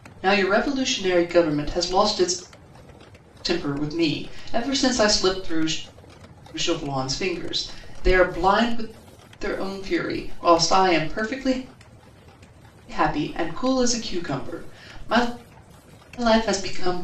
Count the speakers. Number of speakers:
1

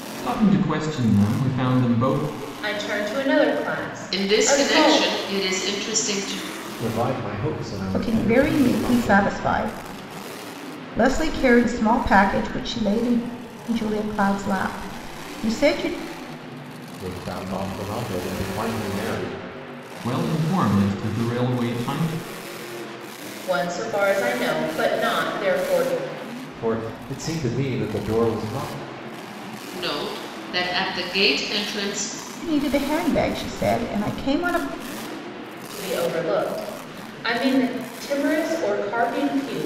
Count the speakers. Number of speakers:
5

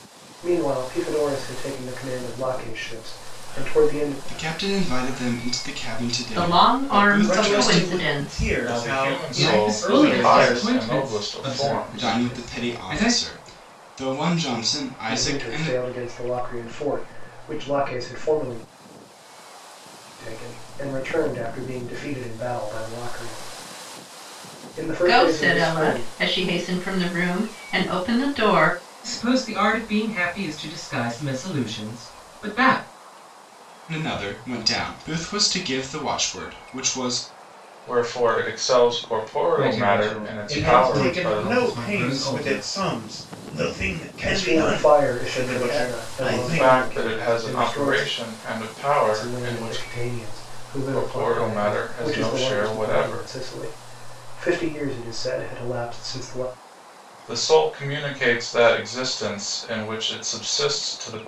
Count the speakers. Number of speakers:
7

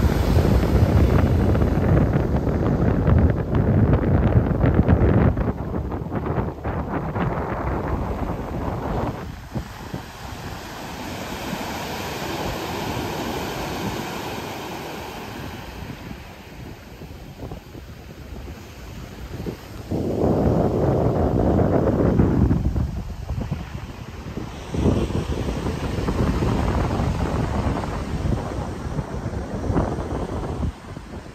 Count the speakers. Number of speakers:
0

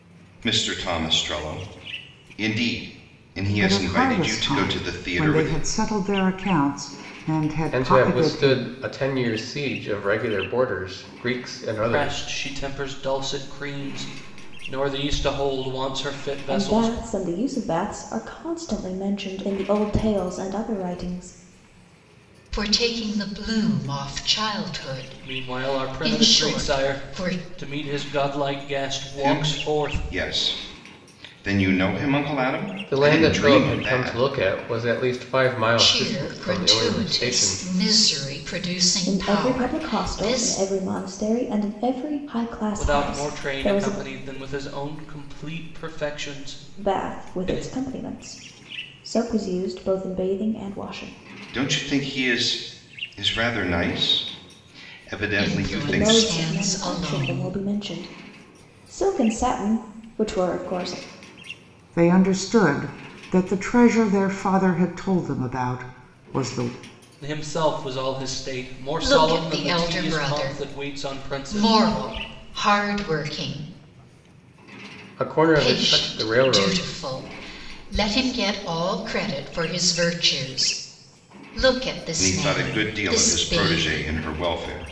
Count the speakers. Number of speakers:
6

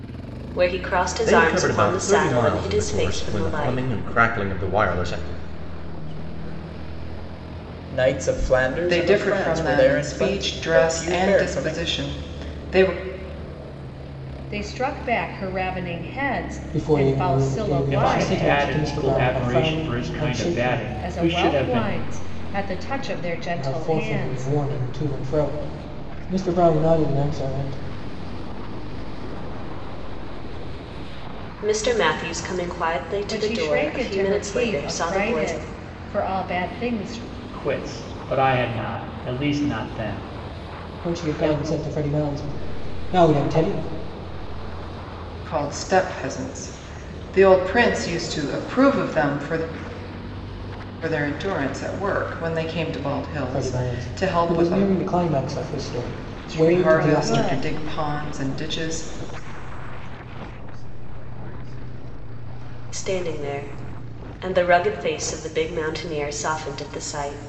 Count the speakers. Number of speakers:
8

